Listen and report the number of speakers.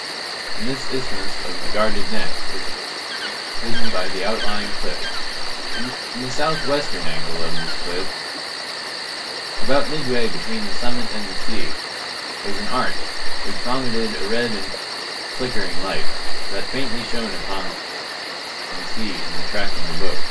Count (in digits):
1